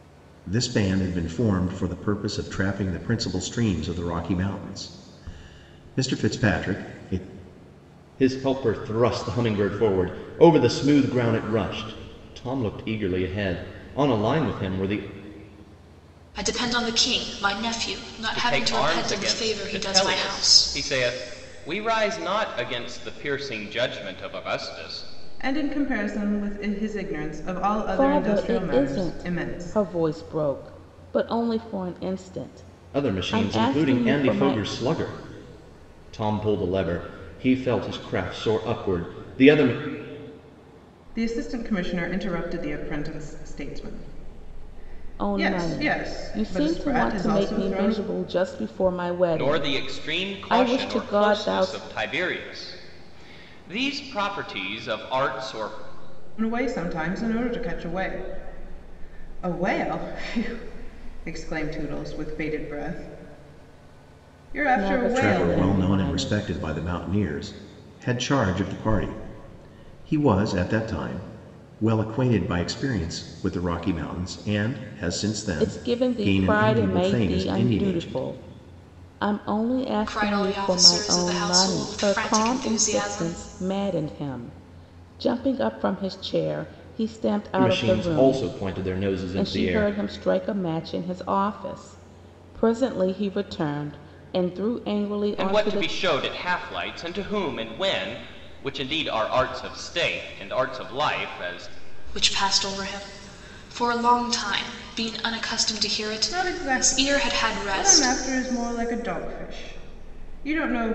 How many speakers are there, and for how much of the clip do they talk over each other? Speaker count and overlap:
six, about 21%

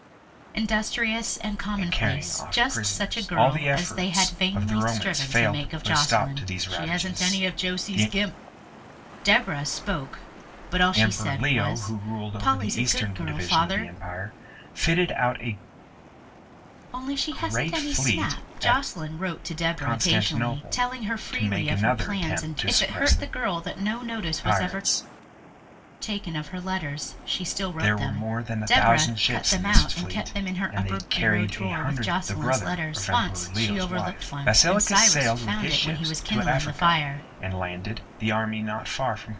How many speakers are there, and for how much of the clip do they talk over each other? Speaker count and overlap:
two, about 60%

